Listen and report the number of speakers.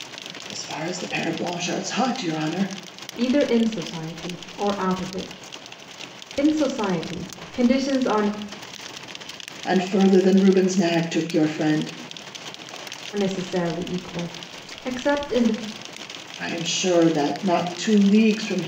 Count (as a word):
two